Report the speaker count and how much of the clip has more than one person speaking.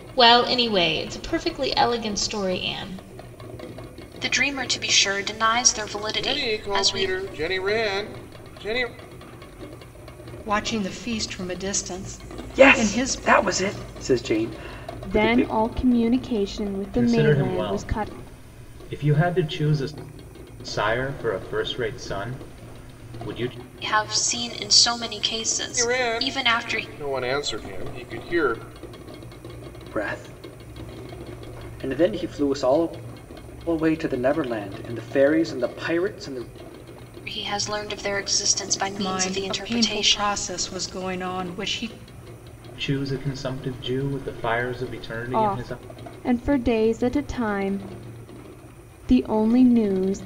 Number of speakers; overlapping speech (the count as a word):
seven, about 13%